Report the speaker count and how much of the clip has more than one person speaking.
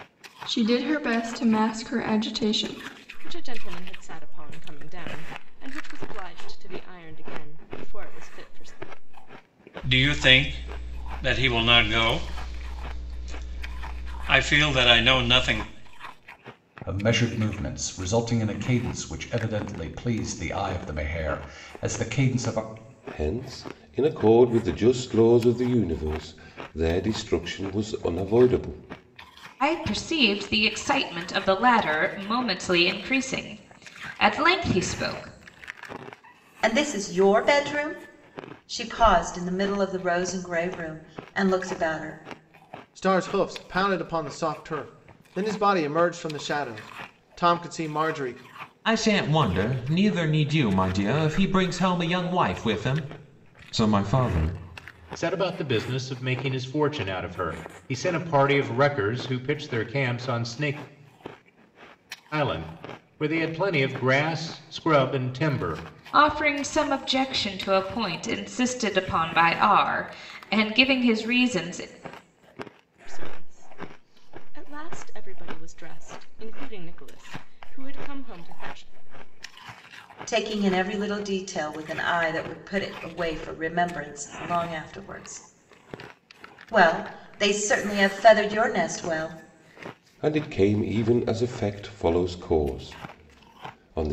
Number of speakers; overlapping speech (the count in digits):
10, no overlap